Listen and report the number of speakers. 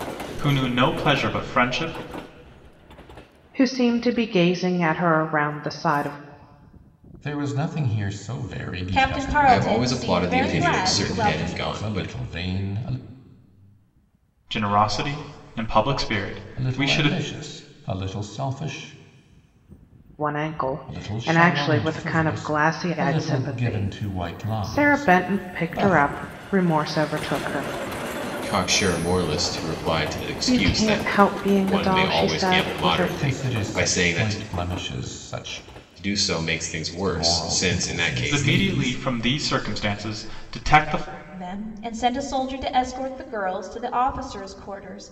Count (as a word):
five